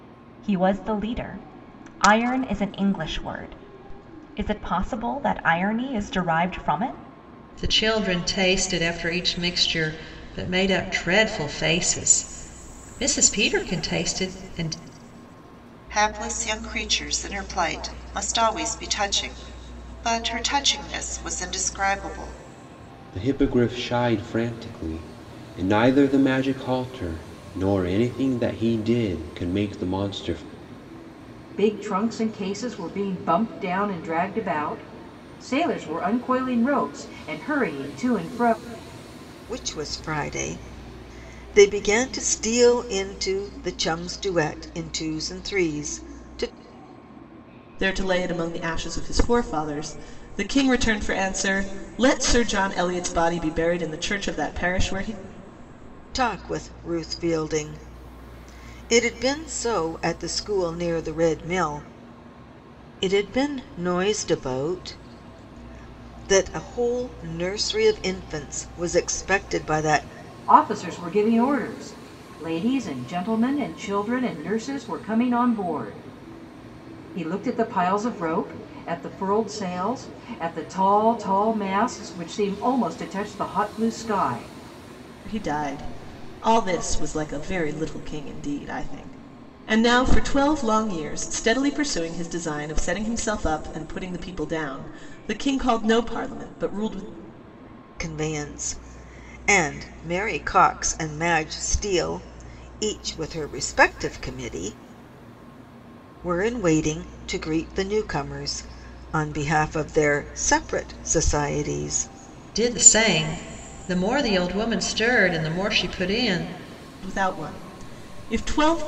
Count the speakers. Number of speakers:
seven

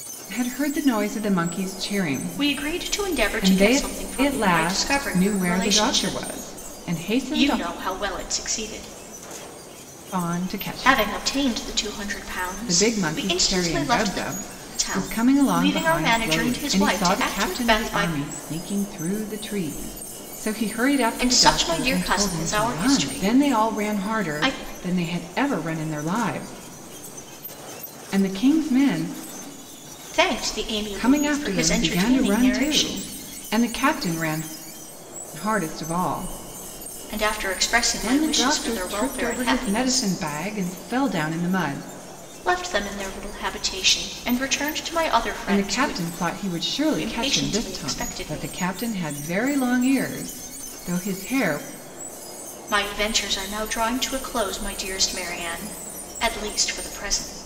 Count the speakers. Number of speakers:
two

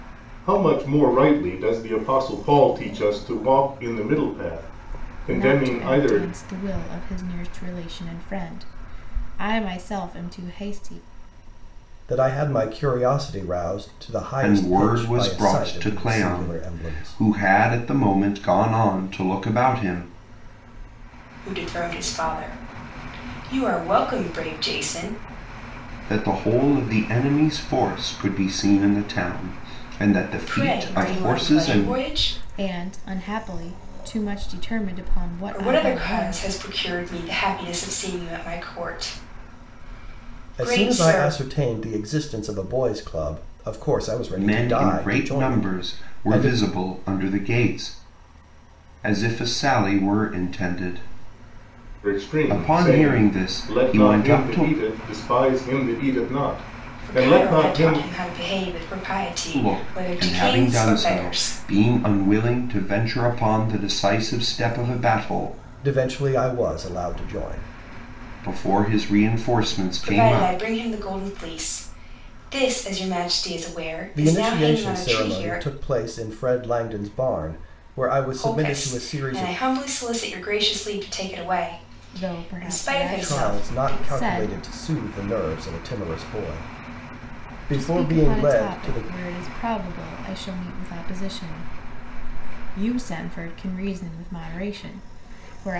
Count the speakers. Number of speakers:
five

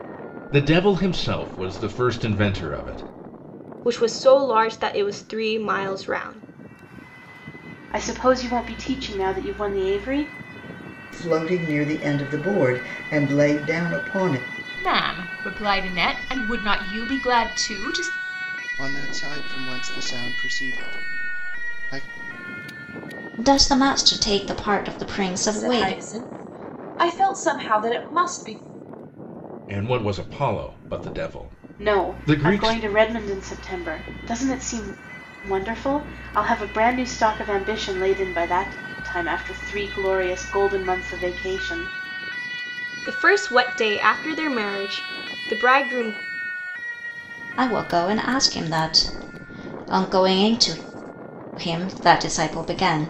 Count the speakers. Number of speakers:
eight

